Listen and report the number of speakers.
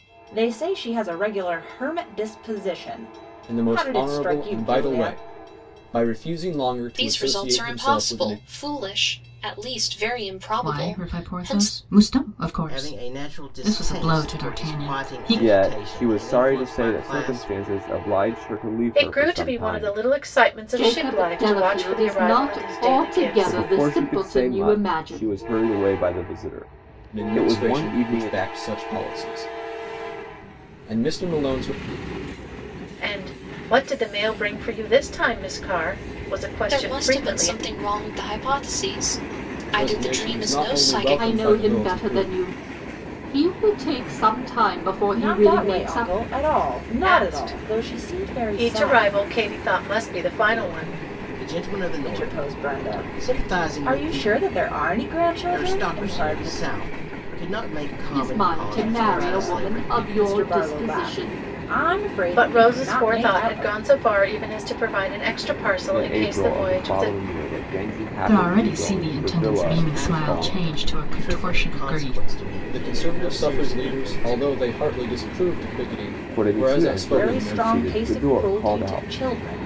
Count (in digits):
8